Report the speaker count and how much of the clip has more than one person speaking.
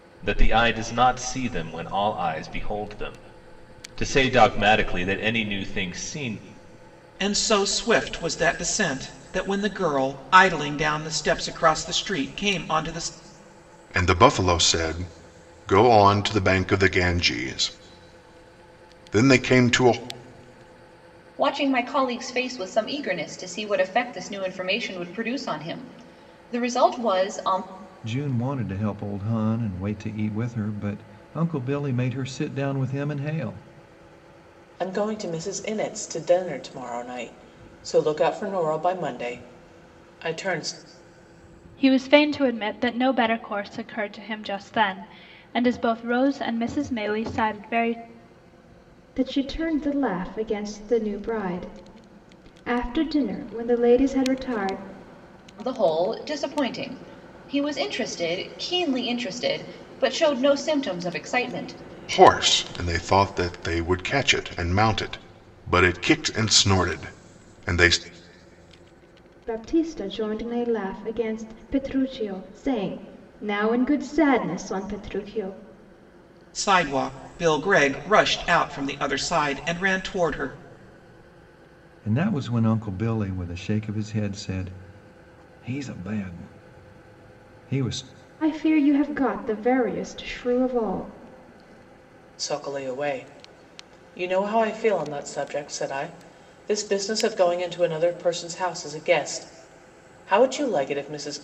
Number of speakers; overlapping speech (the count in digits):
8, no overlap